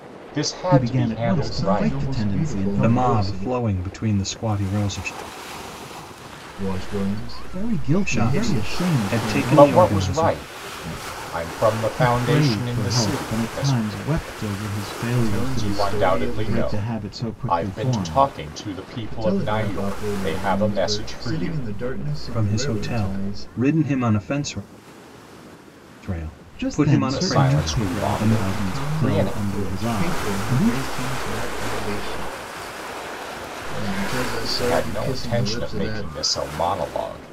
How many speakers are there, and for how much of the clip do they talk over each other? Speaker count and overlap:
4, about 57%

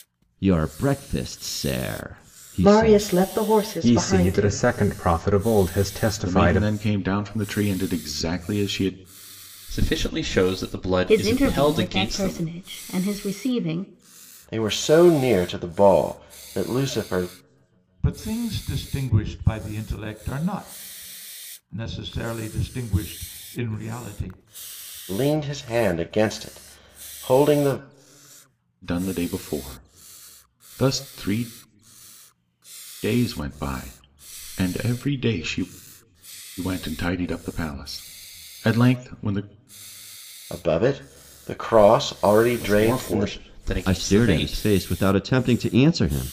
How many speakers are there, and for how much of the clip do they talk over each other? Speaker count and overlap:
8, about 11%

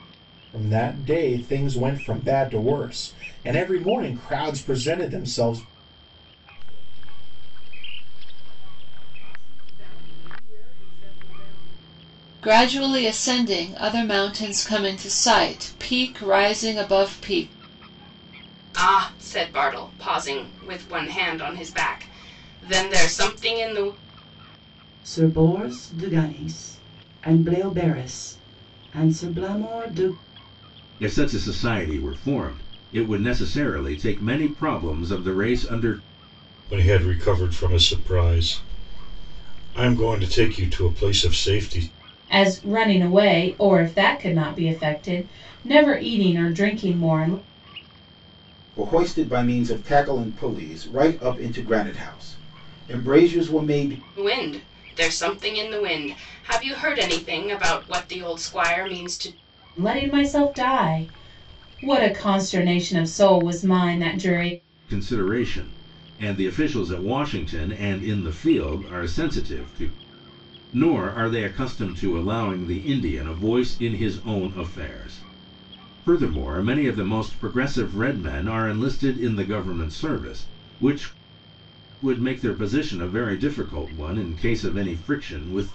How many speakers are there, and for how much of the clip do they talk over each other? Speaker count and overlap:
9, no overlap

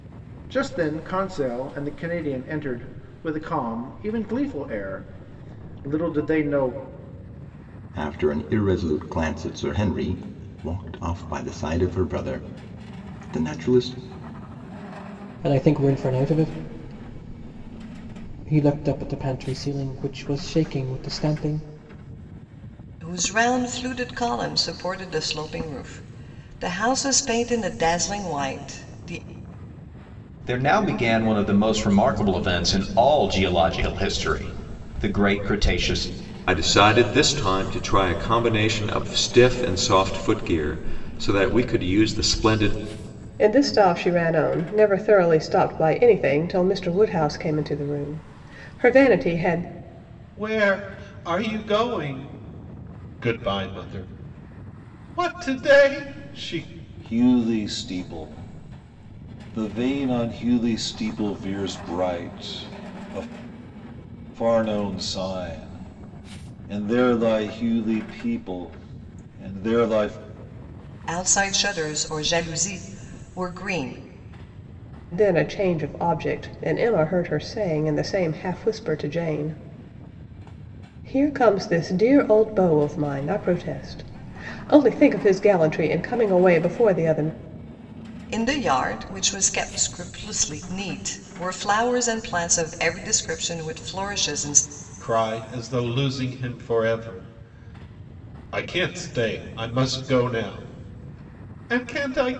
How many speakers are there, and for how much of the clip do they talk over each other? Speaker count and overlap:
9, no overlap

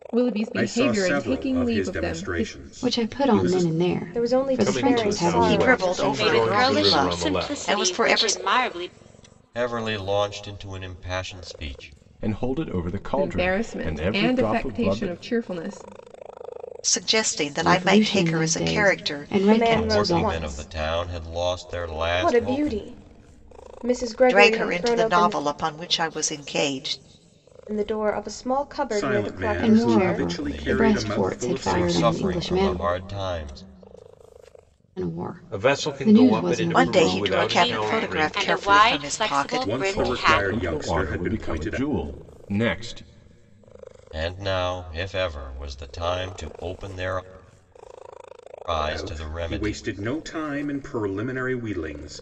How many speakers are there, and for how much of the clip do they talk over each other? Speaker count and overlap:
9, about 49%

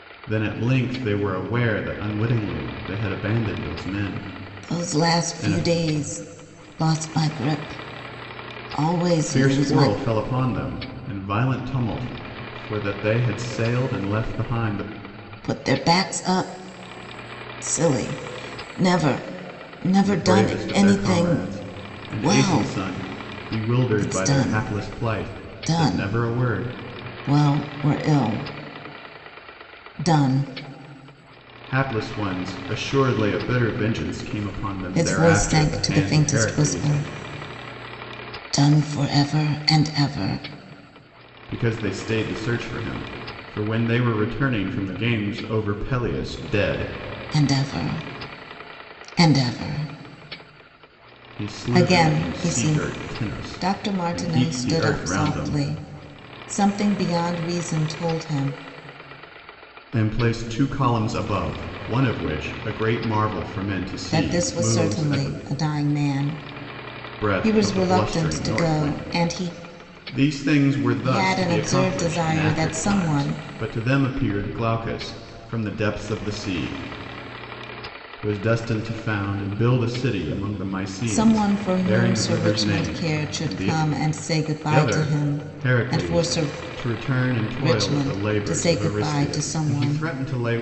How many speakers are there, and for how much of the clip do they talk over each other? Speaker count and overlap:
2, about 29%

